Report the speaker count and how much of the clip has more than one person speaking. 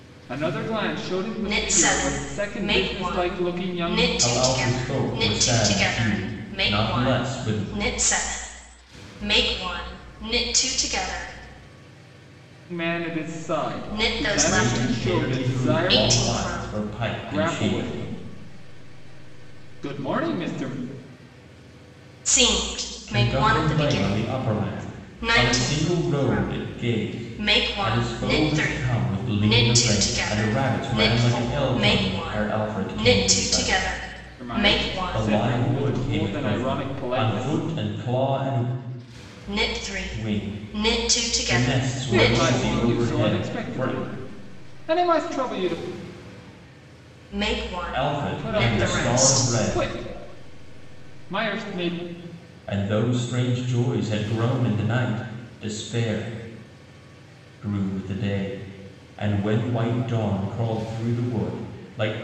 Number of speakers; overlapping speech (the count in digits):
3, about 47%